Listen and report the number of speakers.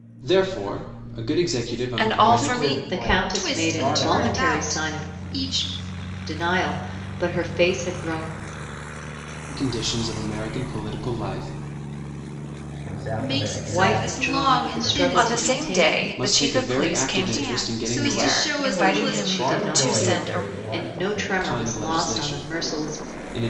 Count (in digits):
5